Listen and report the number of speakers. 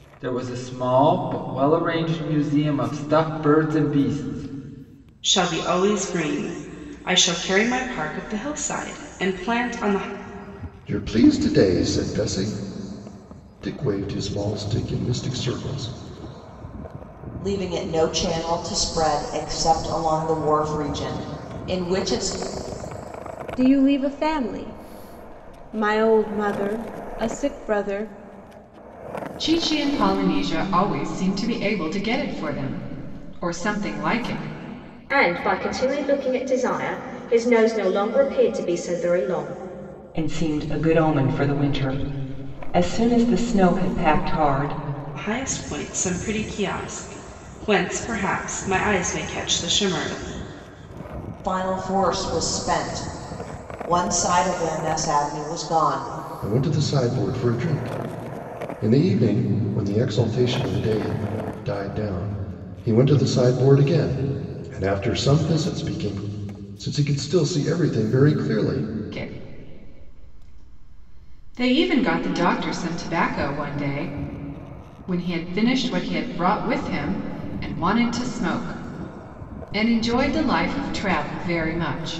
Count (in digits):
8